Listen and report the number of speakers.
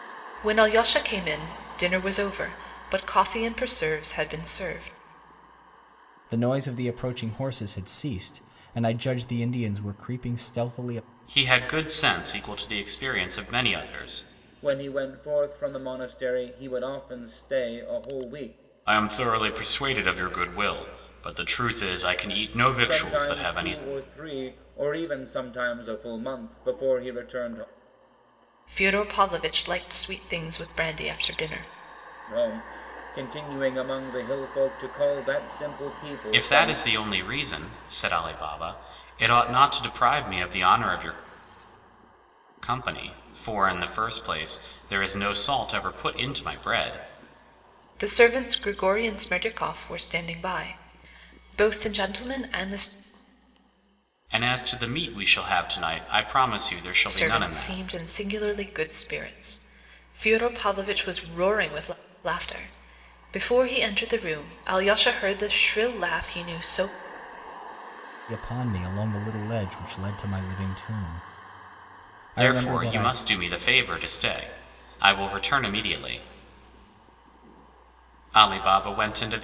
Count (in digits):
4